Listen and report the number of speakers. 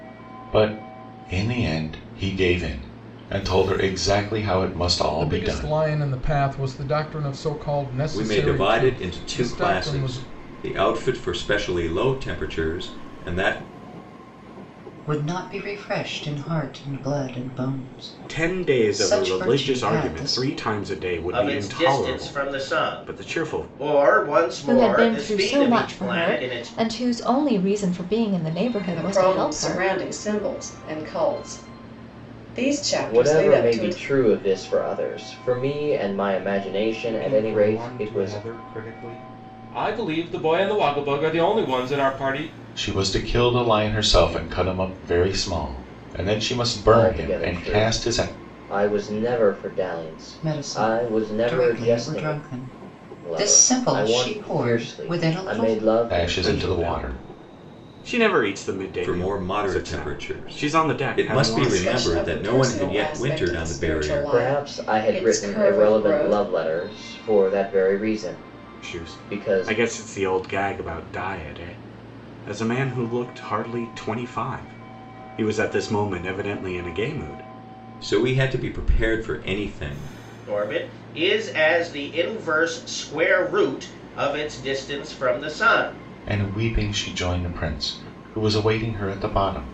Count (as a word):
ten